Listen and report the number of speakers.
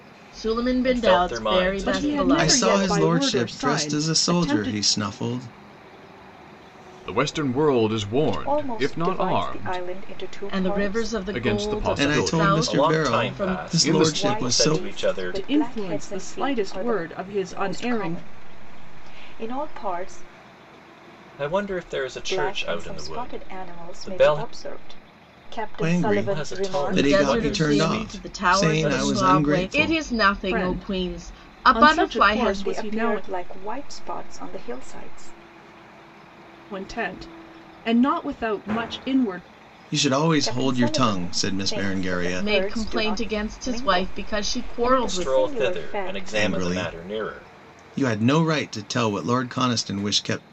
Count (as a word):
six